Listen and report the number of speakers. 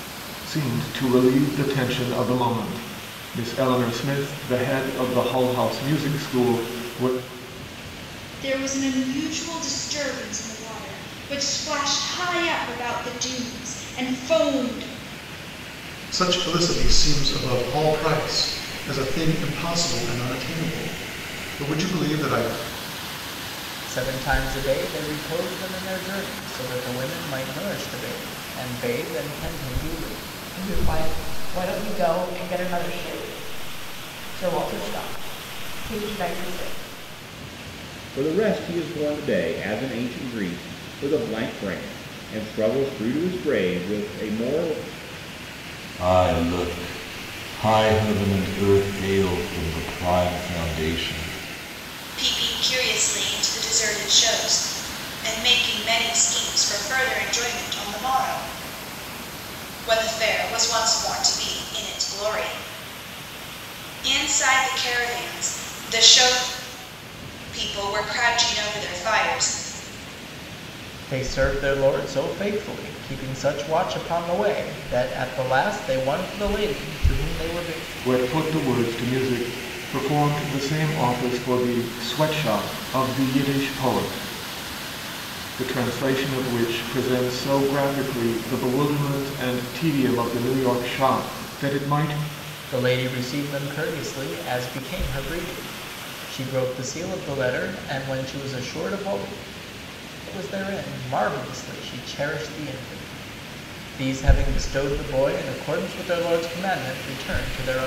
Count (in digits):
8